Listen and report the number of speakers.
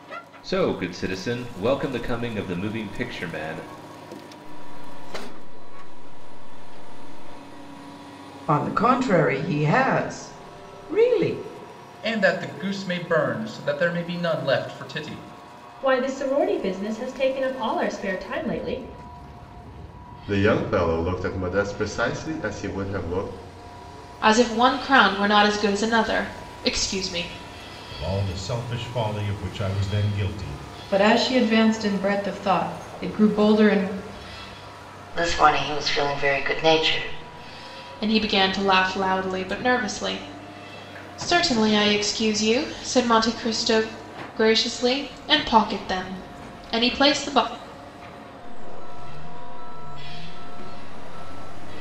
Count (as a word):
ten